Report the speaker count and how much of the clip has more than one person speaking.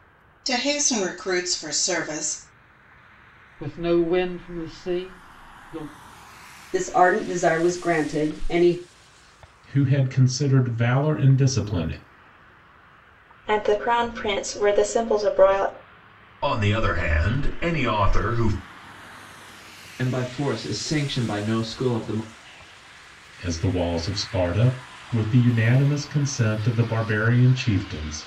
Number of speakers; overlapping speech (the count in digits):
7, no overlap